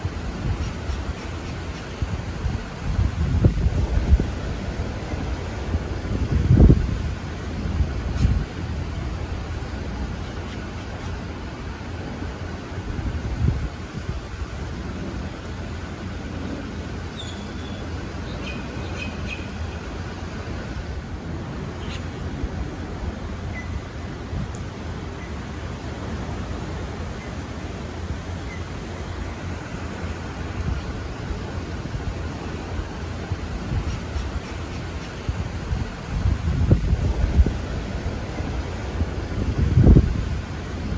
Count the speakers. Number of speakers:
zero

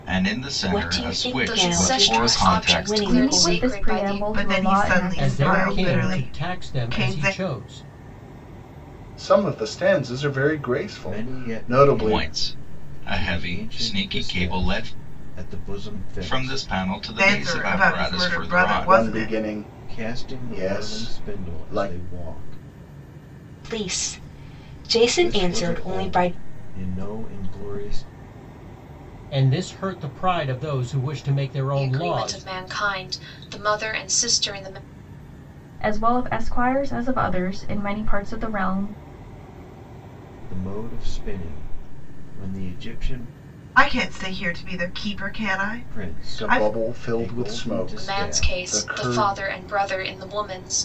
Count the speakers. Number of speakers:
eight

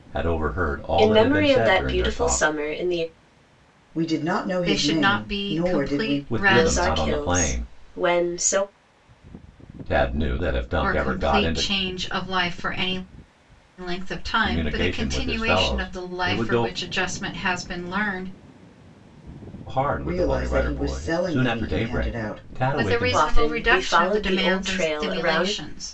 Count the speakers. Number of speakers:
four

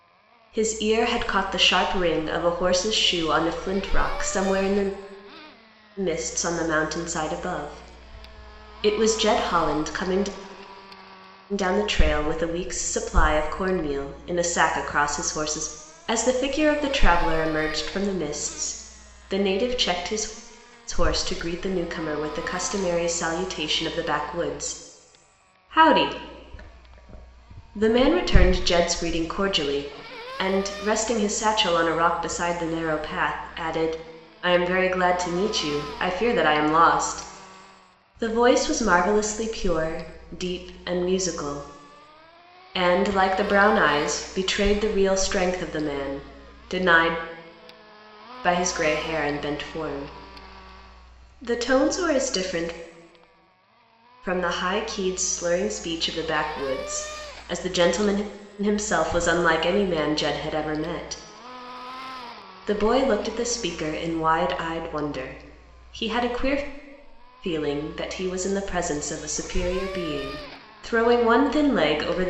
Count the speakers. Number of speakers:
one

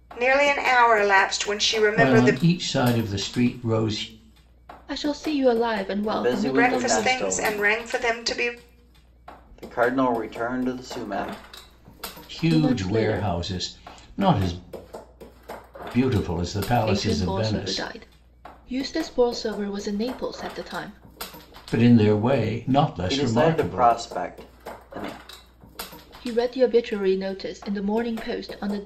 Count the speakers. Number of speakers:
four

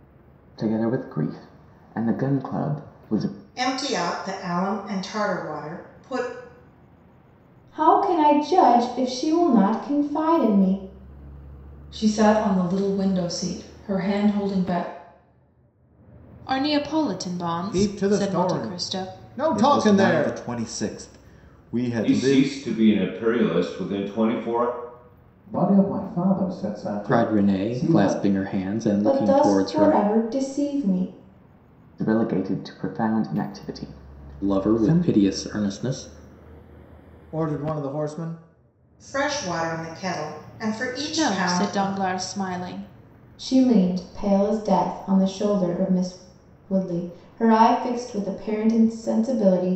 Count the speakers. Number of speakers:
ten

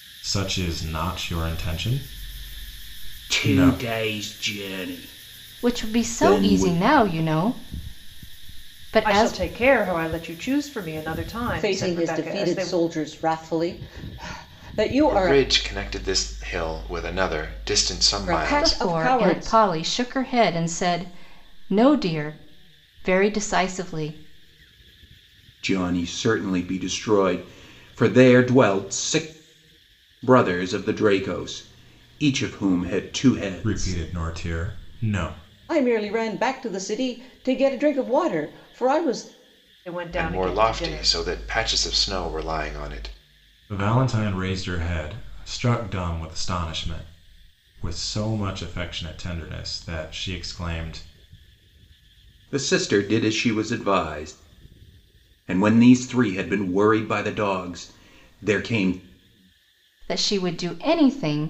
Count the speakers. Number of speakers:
six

